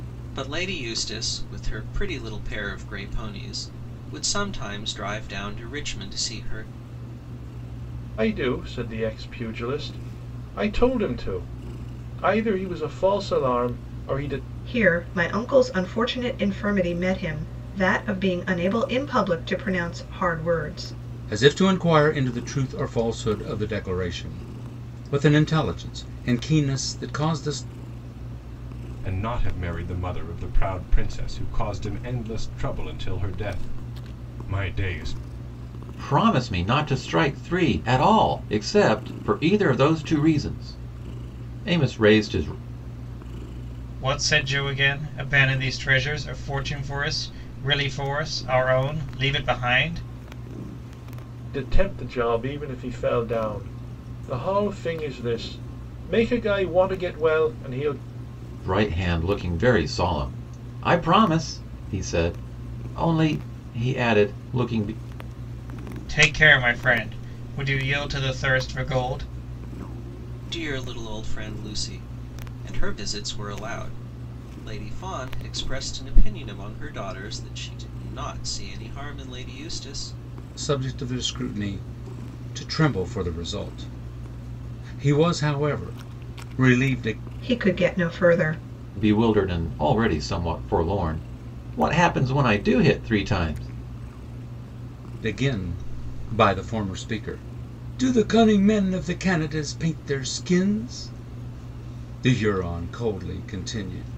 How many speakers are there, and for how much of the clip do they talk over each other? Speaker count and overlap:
seven, no overlap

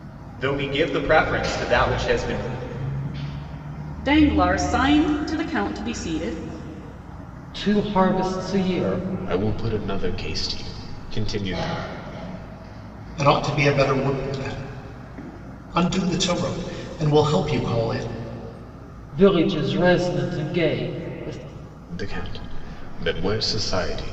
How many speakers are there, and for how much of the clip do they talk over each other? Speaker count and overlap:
five, no overlap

